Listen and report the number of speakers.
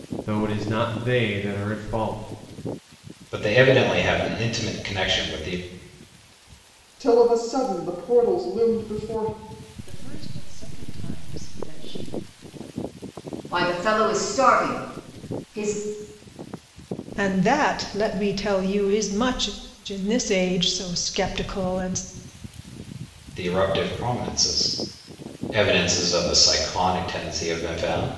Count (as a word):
six